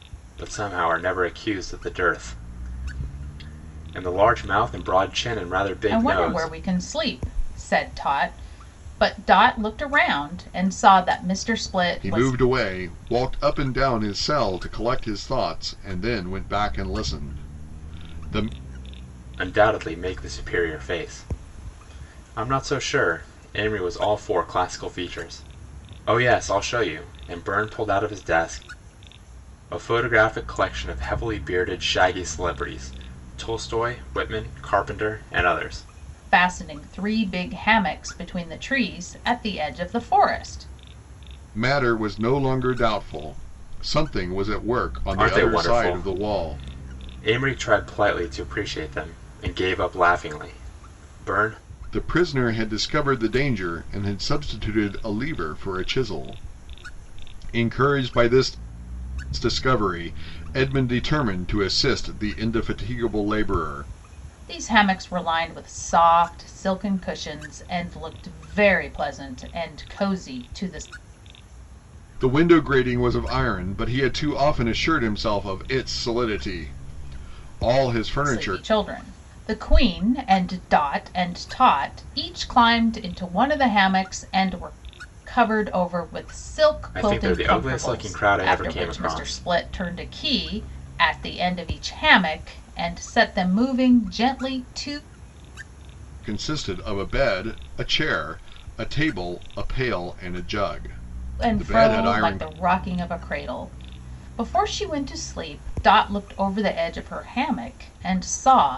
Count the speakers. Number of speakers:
3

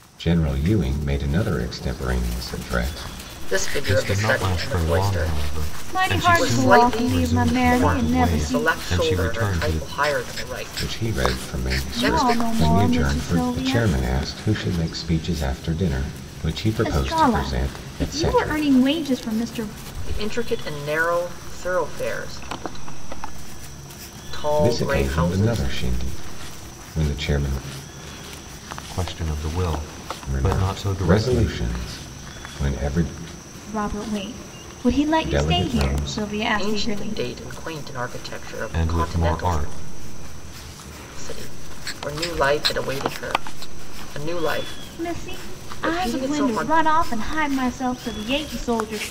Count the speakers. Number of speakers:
4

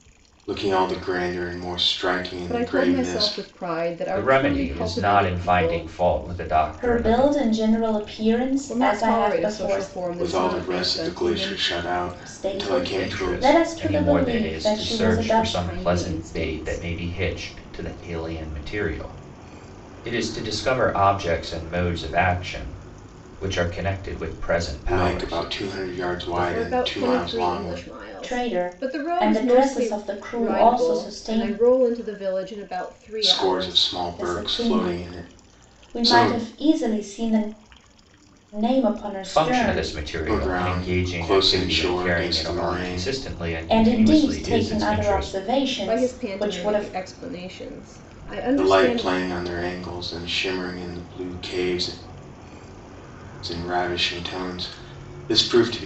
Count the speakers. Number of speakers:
4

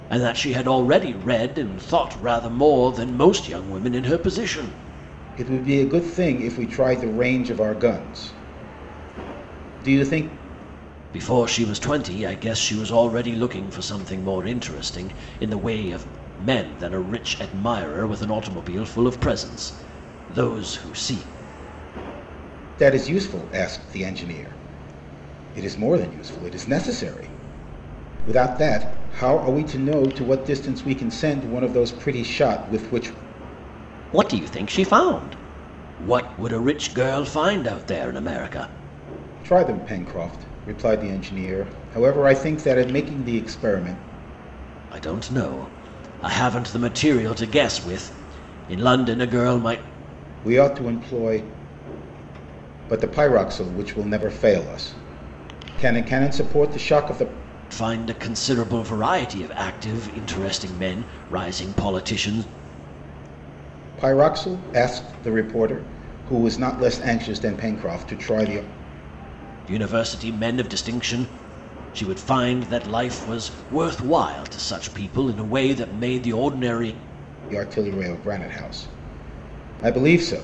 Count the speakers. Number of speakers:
2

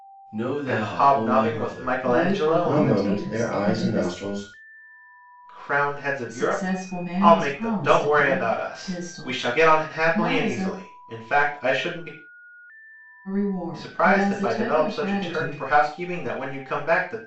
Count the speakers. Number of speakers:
4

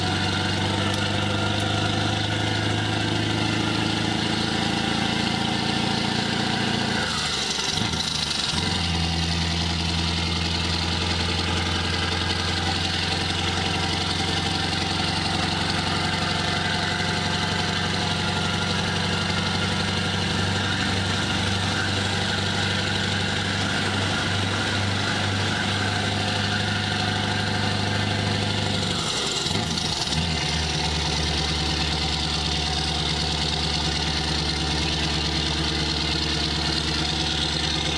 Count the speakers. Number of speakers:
0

